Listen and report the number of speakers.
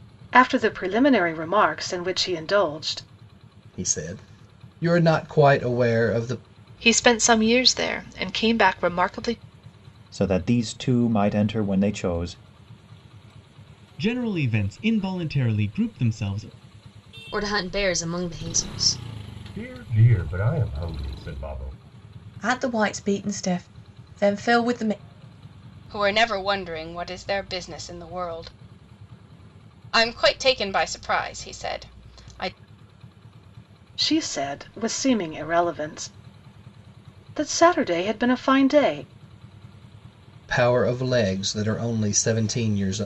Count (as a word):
nine